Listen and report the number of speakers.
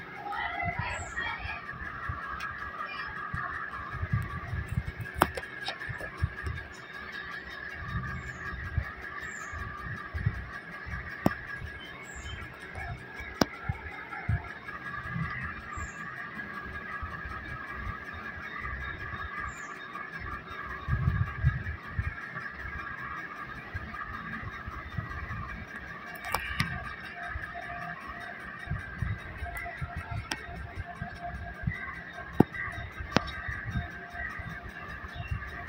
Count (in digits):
0